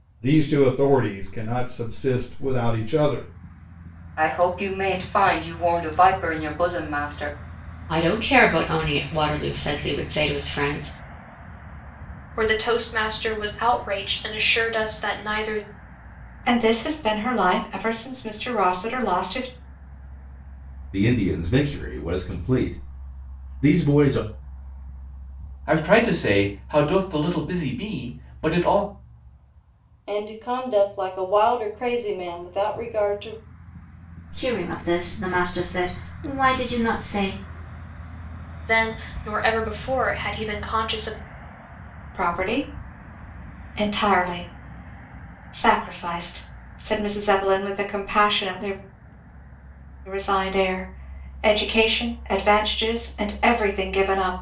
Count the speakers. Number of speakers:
9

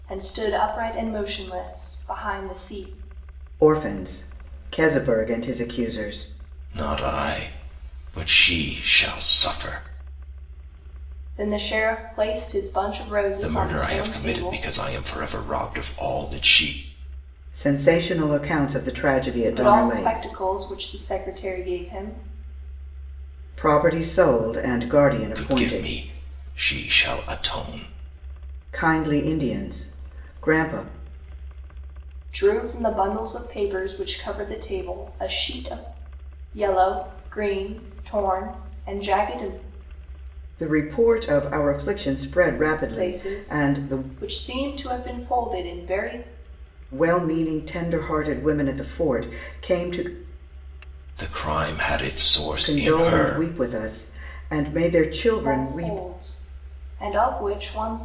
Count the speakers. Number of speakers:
3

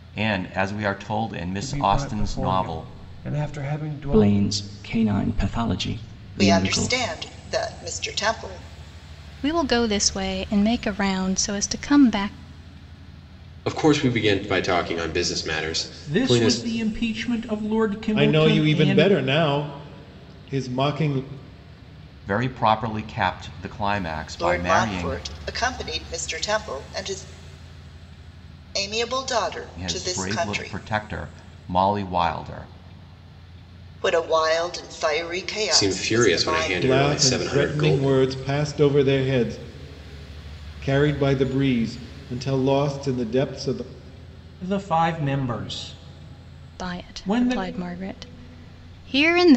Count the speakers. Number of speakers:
8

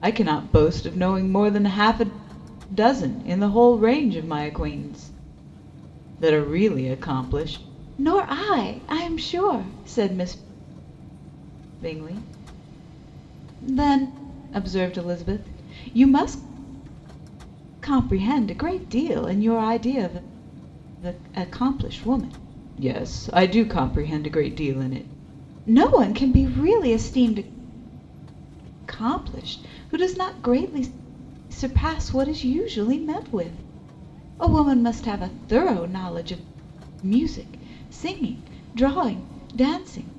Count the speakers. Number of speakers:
1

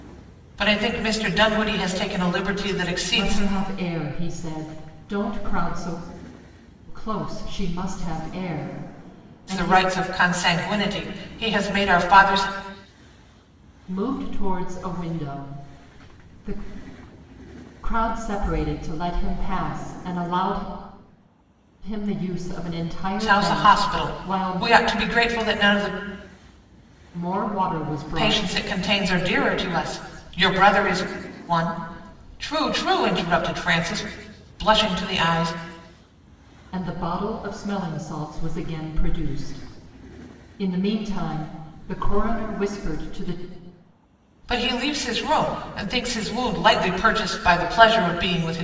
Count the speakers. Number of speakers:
2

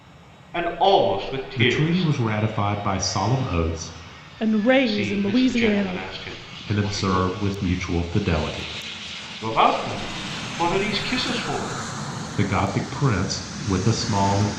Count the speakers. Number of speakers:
3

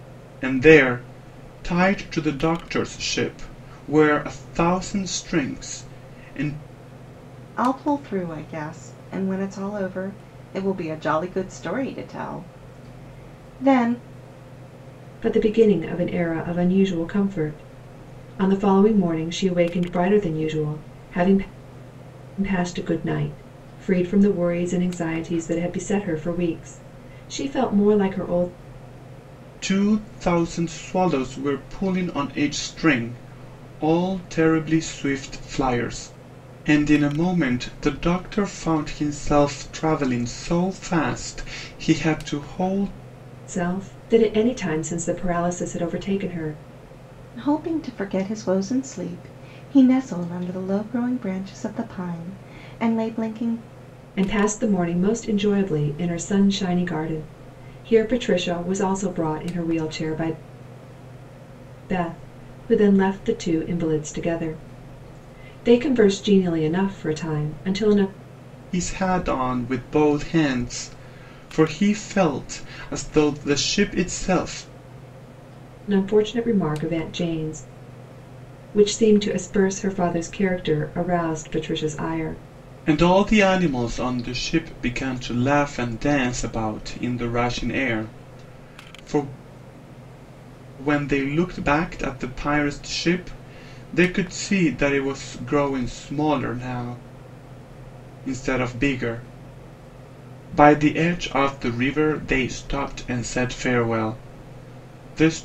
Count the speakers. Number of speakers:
3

